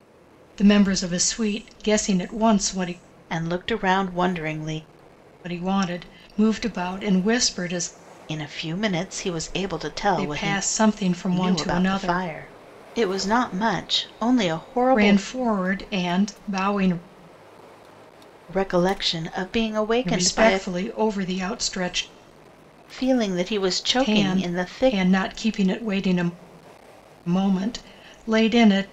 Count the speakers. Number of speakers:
2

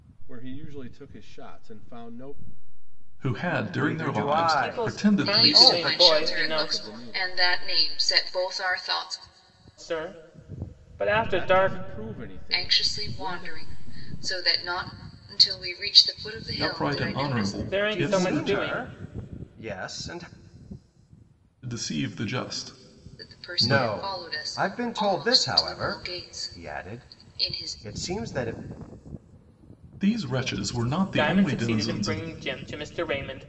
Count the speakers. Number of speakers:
5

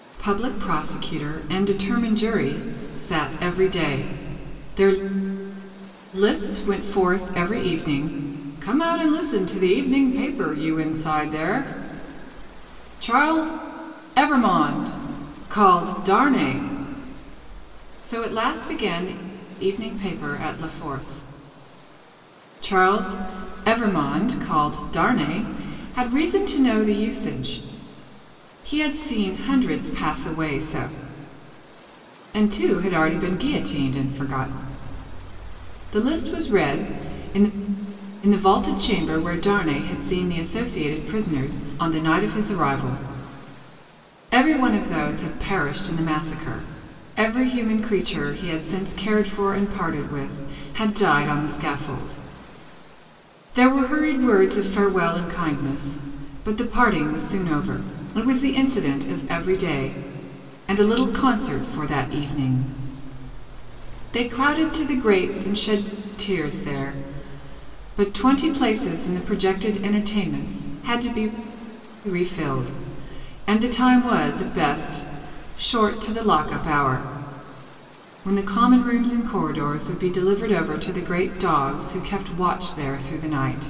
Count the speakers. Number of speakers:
1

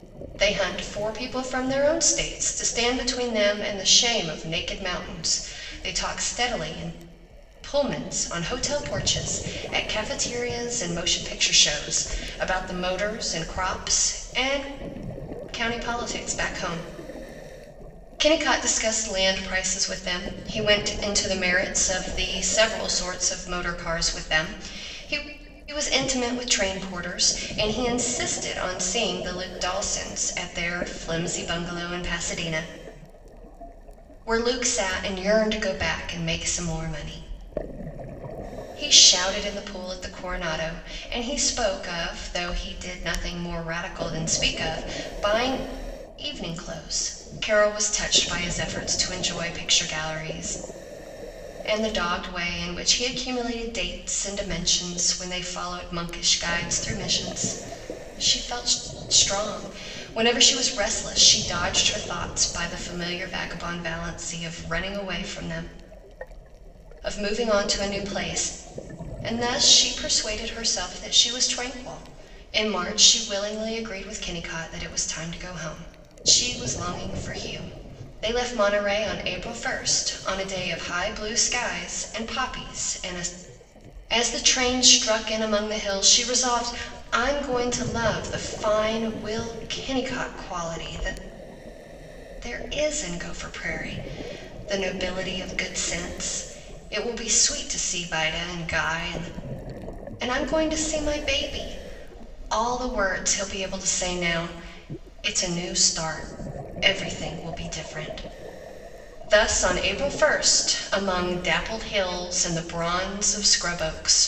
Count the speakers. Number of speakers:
1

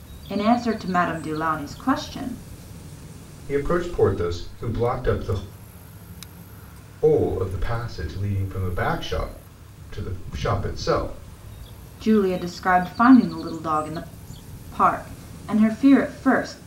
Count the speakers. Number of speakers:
2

